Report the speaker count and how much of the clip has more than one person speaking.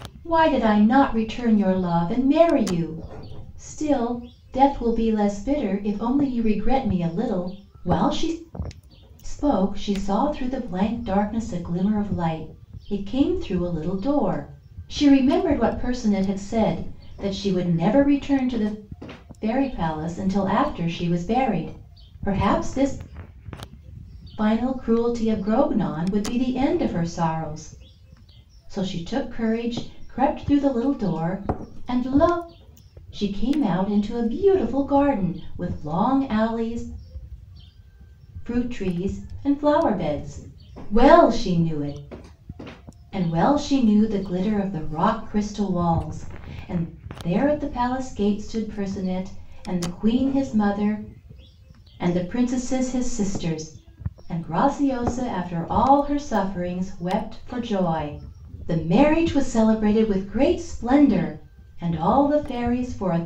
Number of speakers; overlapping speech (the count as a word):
one, no overlap